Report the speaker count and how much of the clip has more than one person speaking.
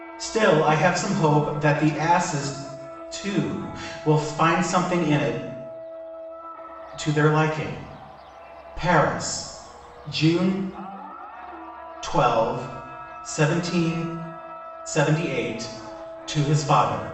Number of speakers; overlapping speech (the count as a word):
one, no overlap